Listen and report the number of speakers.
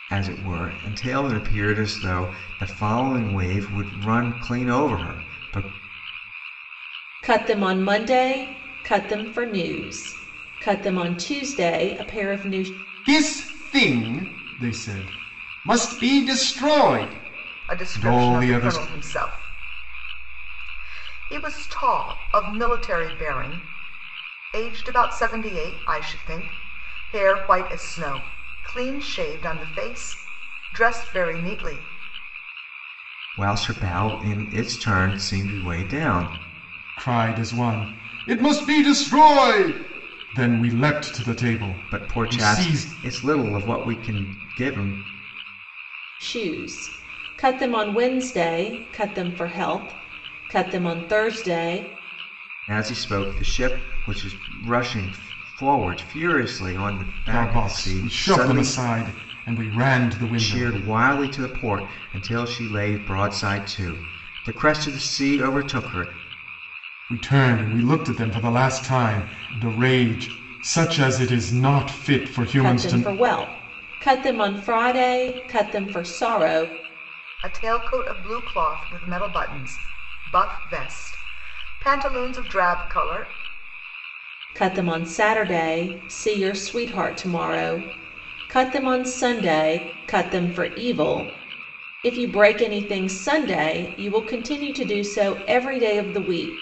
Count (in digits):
4